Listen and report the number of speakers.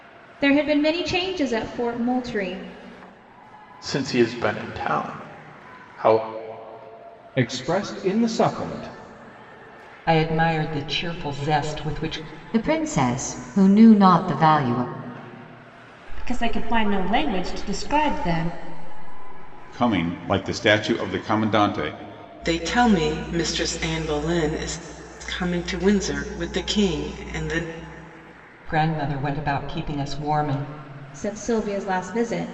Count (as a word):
eight